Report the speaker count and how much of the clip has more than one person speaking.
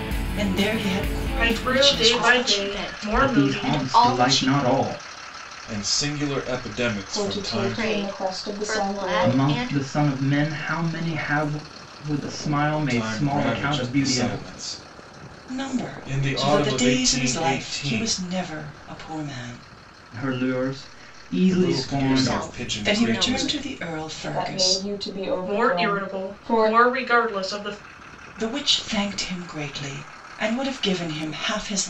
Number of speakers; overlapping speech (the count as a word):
six, about 45%